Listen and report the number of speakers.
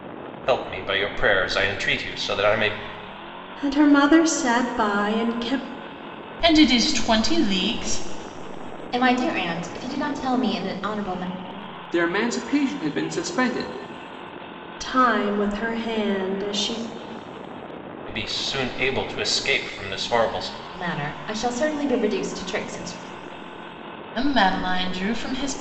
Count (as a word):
five